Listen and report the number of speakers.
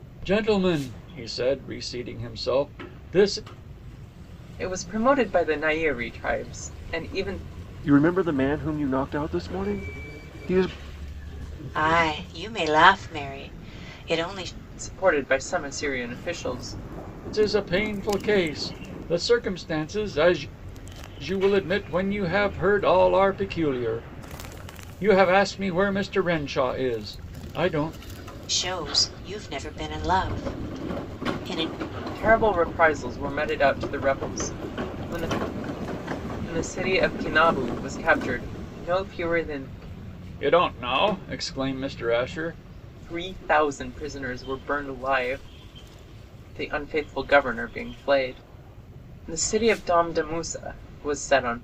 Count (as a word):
four